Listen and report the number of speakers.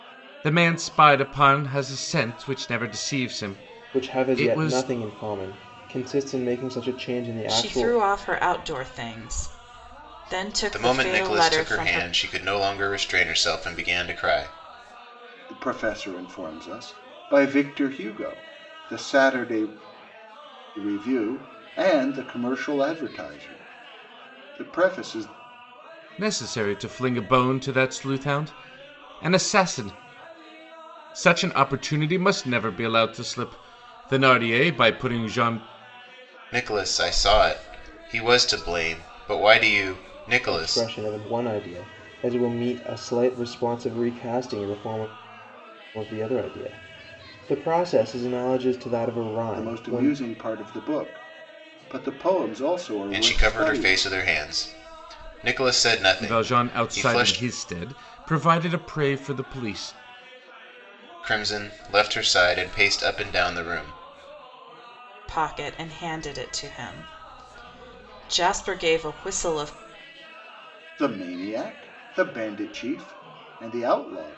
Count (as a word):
five